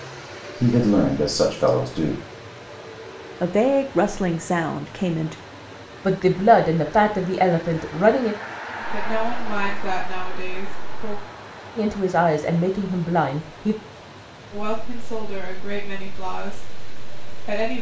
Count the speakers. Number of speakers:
4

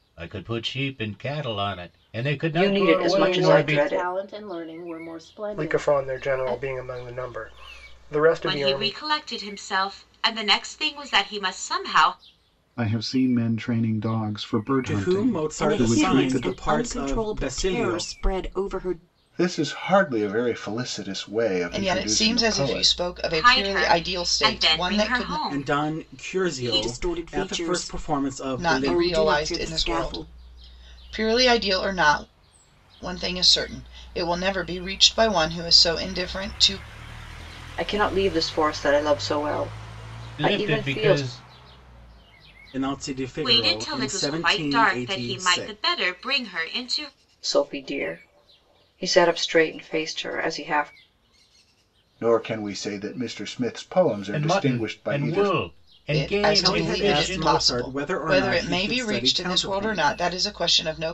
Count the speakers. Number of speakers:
10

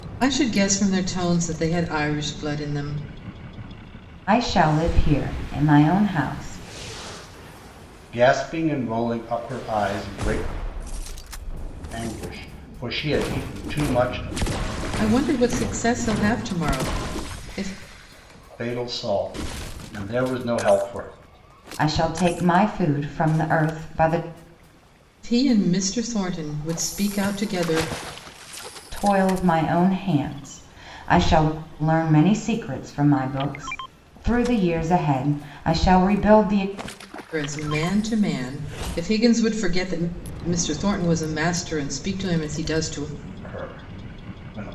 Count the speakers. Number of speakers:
3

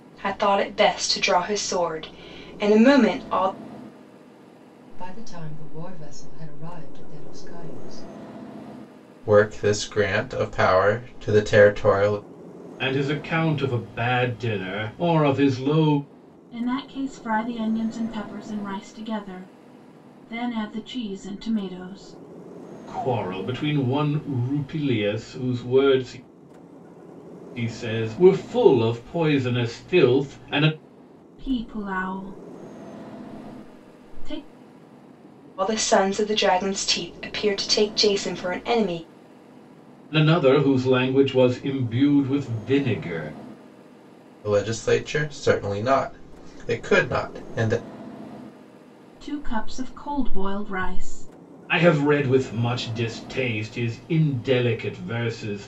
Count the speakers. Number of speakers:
5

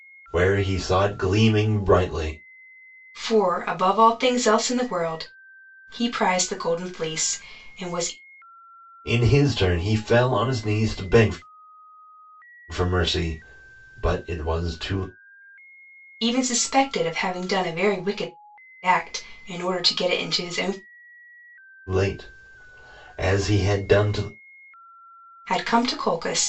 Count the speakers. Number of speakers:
2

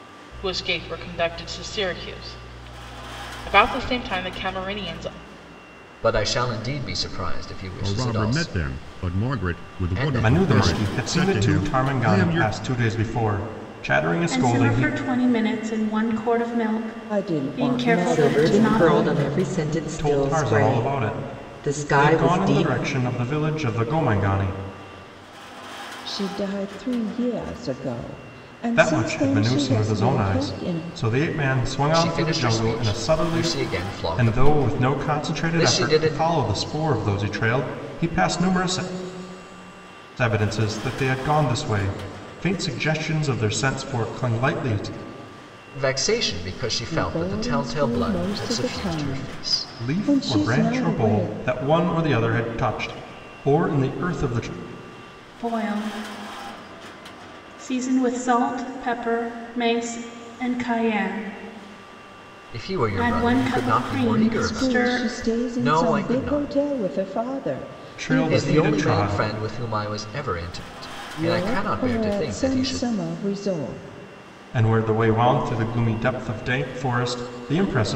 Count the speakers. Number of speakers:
7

